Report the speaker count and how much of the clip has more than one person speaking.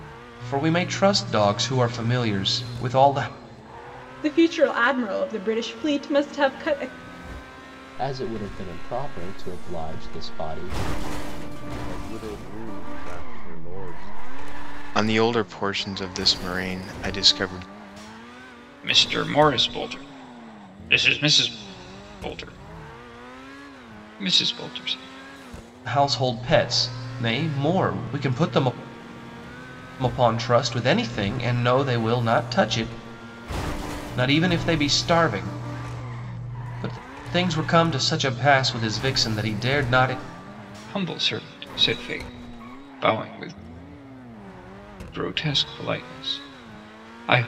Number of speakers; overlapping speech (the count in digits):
6, no overlap